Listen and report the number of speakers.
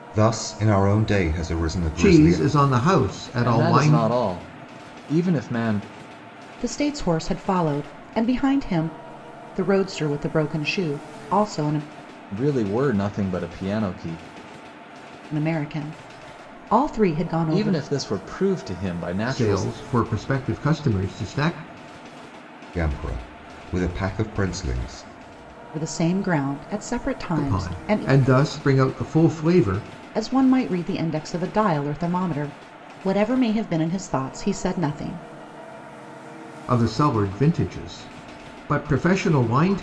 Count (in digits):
4